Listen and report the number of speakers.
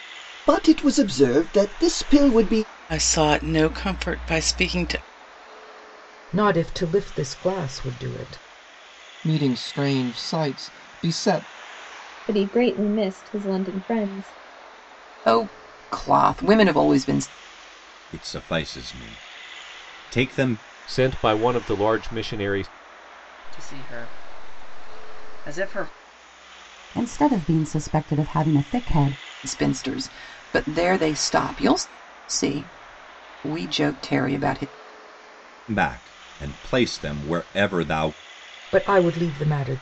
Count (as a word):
ten